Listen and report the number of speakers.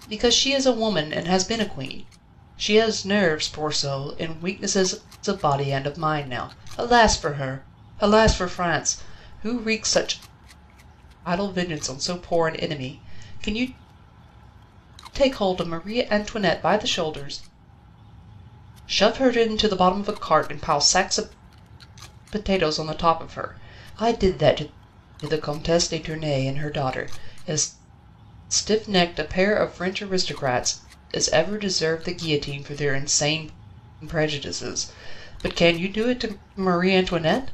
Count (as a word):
one